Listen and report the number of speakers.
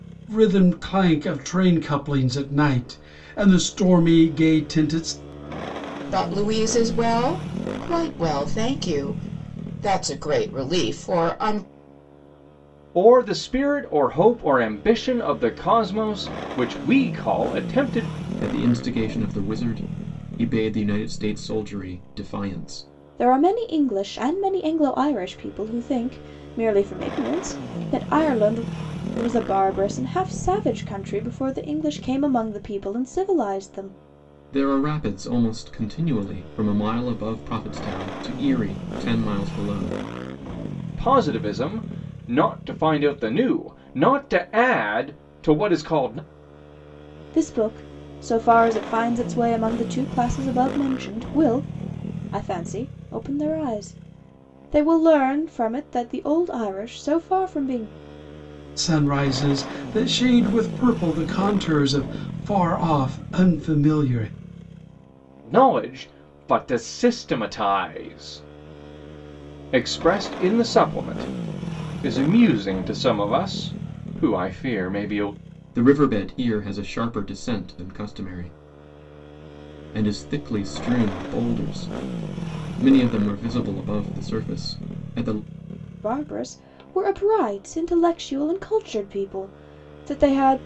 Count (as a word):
five